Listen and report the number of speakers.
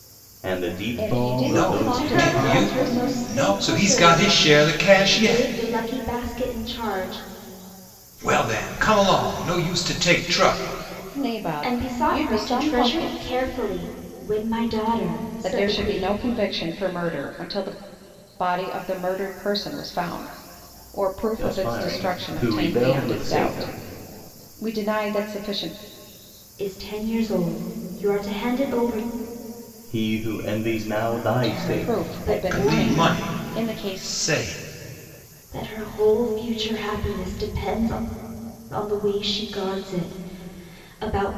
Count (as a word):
four